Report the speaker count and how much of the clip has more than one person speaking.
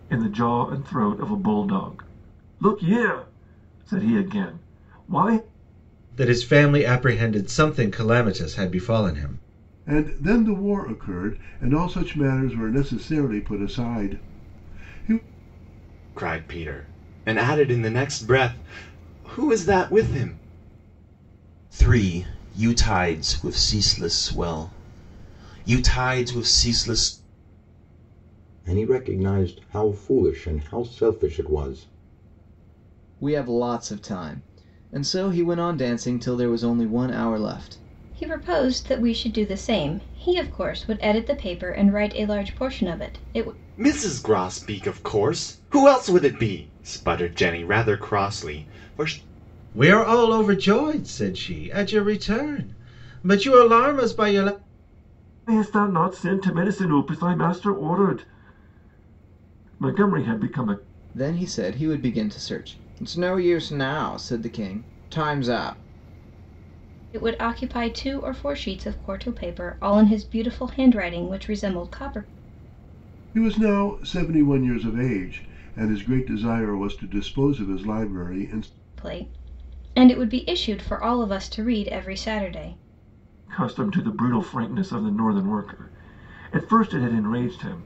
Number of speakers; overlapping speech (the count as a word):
eight, no overlap